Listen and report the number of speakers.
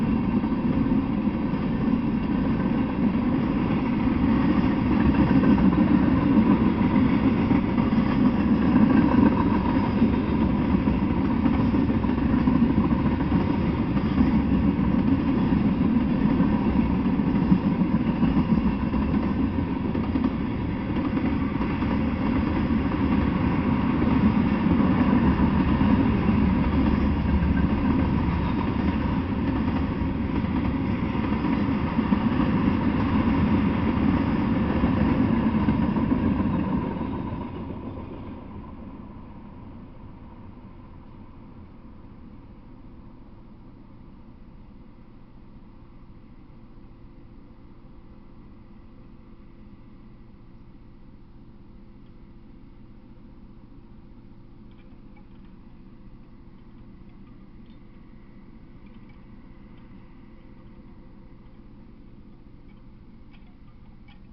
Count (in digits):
0